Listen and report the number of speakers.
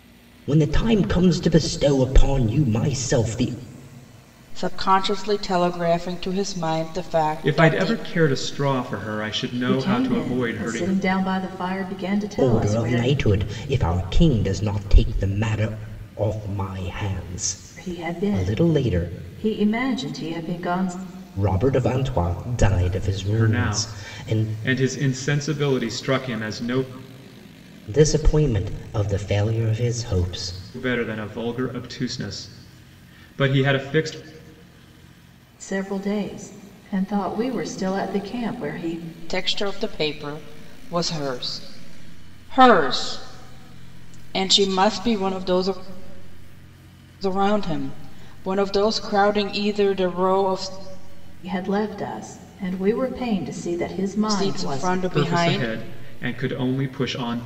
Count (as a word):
four